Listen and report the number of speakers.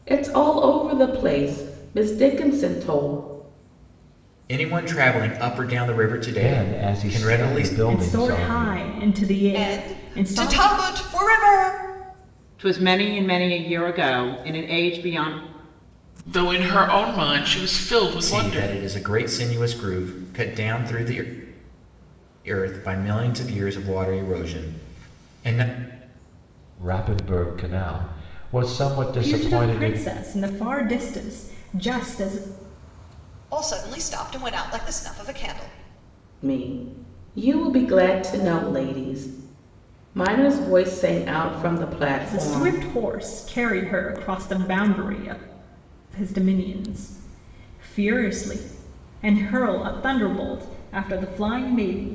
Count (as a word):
seven